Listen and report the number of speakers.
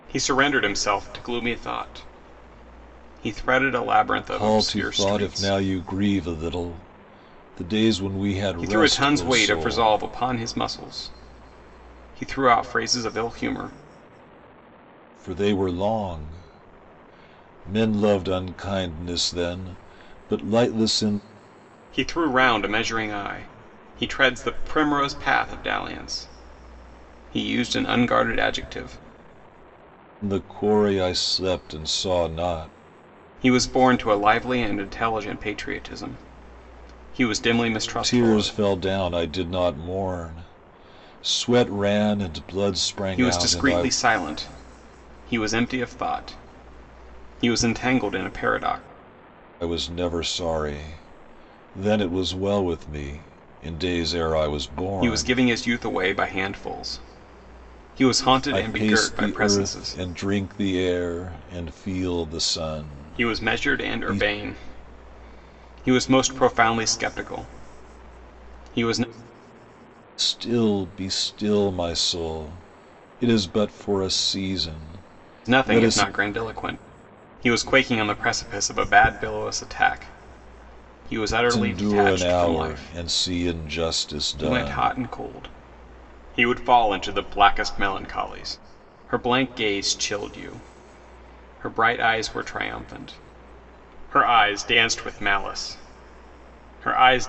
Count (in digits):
2